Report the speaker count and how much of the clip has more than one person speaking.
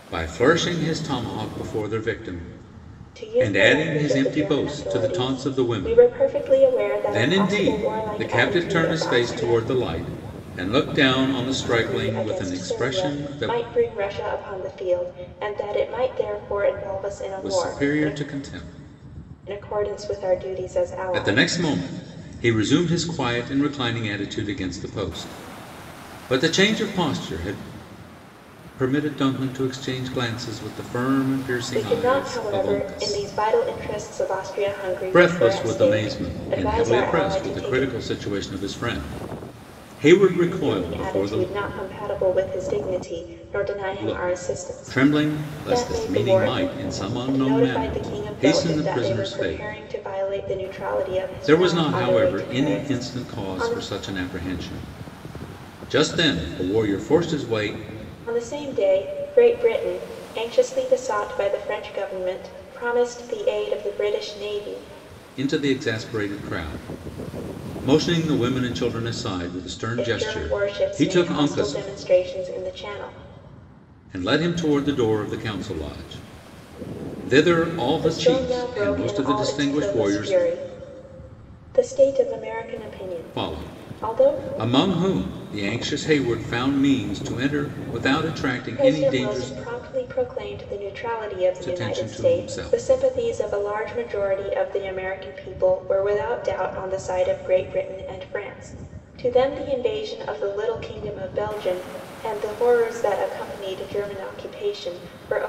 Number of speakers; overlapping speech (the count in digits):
2, about 28%